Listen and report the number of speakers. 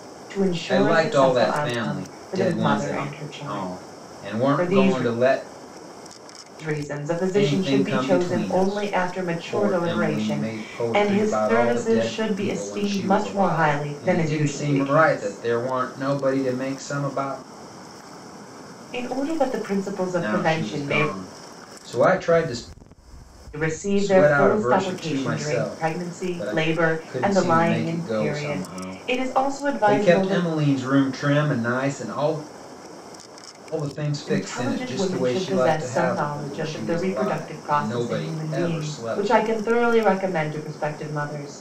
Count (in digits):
2